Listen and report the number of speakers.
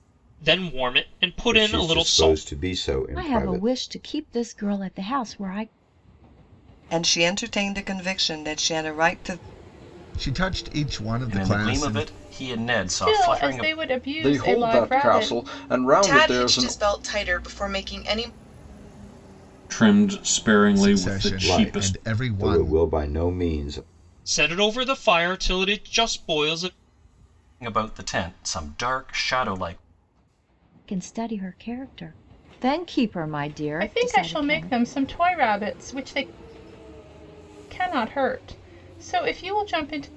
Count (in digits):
10